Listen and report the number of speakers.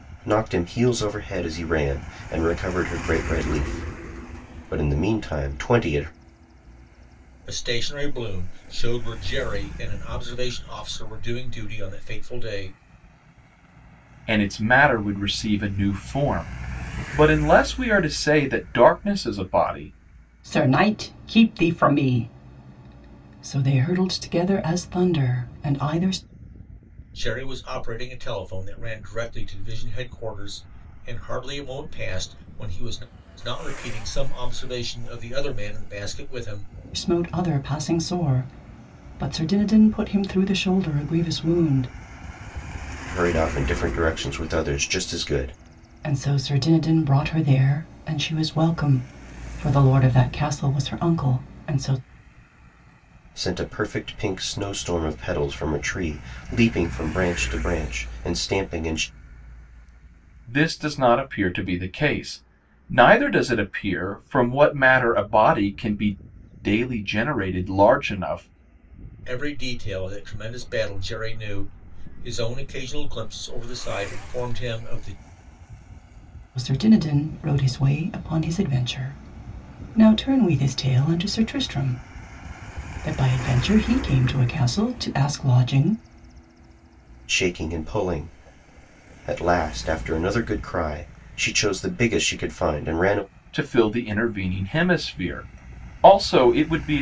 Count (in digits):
4